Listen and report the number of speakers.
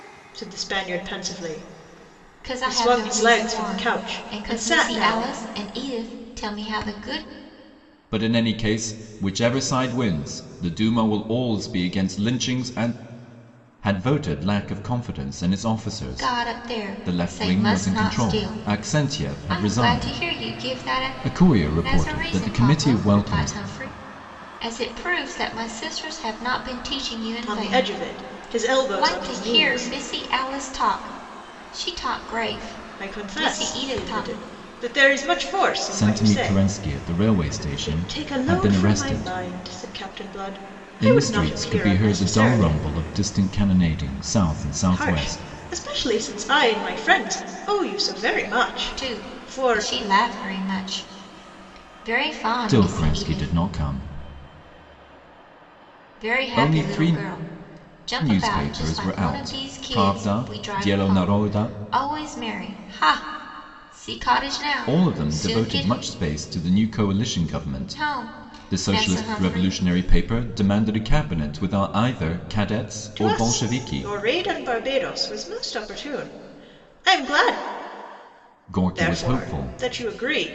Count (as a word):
three